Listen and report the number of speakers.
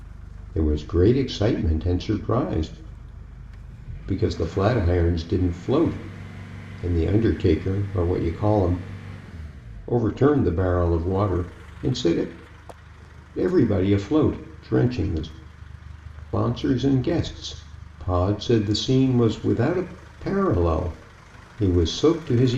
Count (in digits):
1